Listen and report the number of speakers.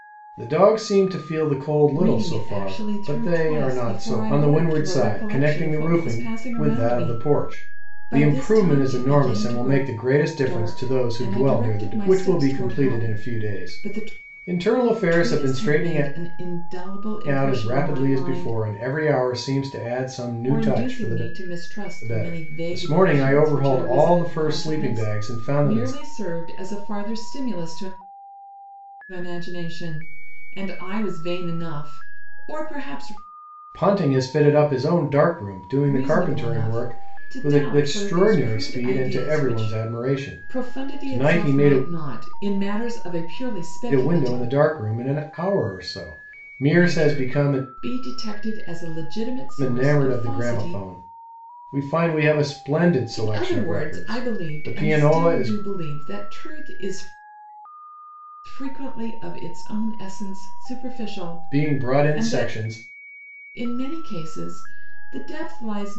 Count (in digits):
2